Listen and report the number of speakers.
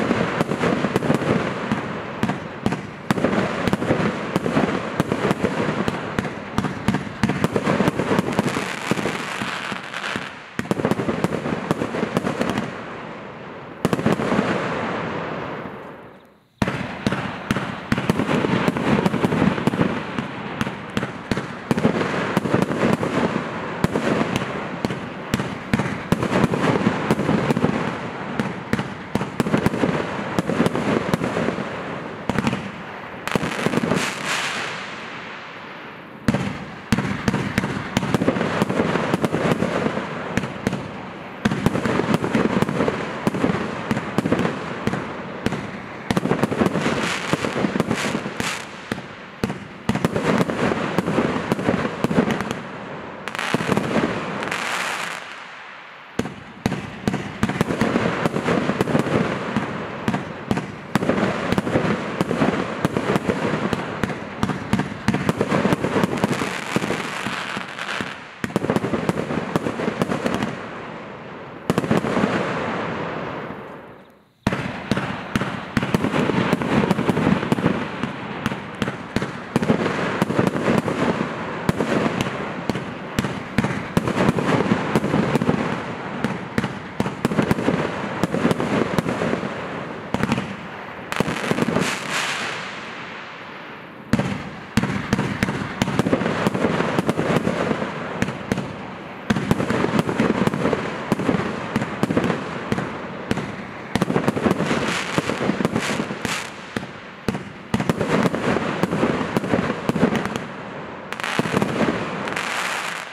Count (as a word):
zero